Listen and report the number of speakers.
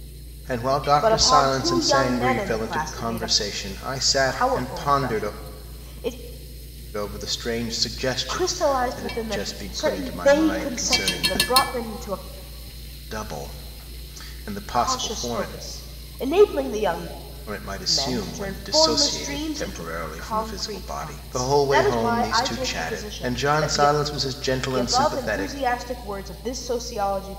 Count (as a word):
two